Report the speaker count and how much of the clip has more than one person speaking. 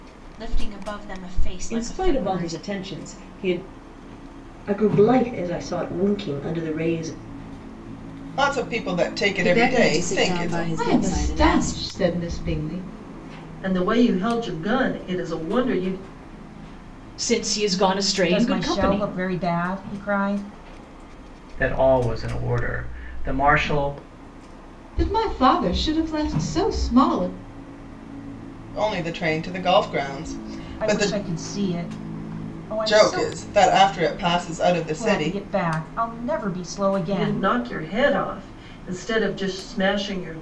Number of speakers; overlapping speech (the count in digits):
10, about 14%